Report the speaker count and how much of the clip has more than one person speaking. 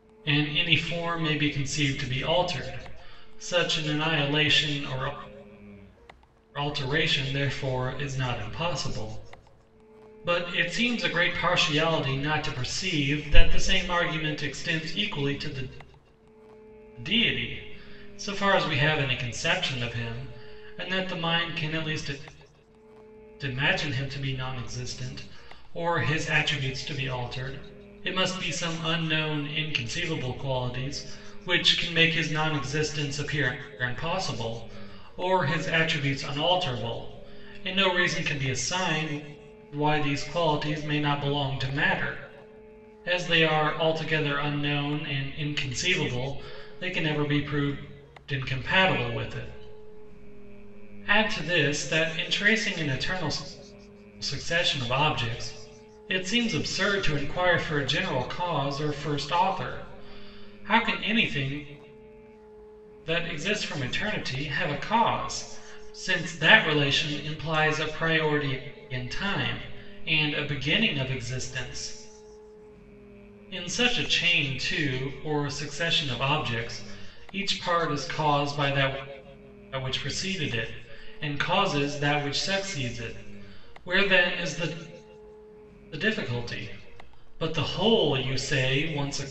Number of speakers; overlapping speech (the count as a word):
one, no overlap